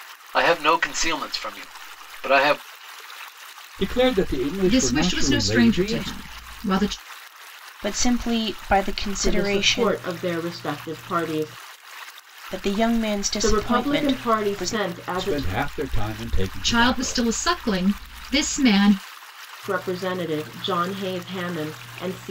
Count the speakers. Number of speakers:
five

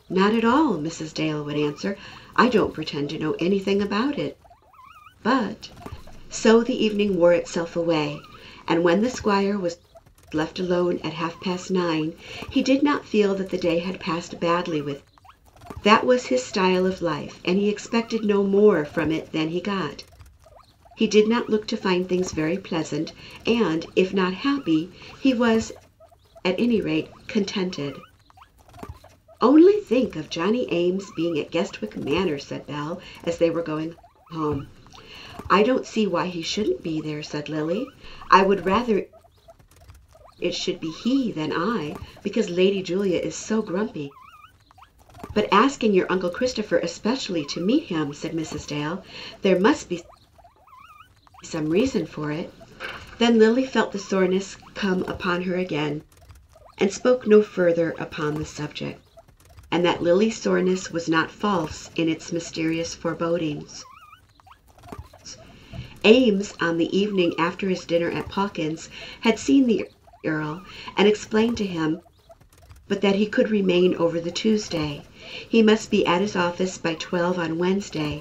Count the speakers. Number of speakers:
one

